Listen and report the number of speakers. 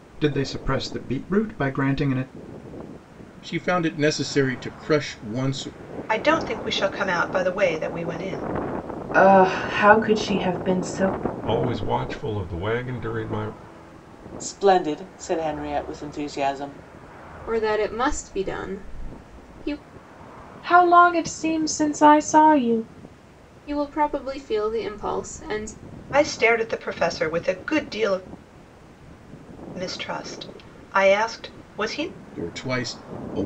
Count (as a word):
eight